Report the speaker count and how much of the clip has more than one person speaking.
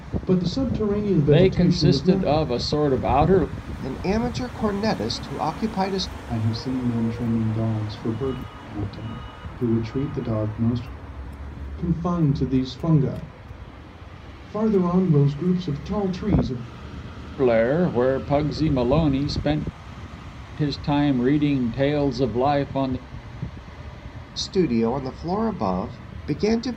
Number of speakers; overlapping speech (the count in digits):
4, about 4%